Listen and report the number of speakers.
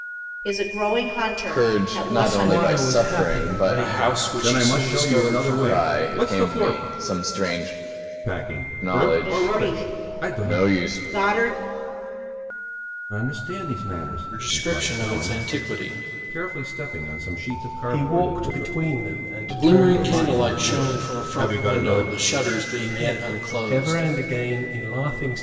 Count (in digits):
5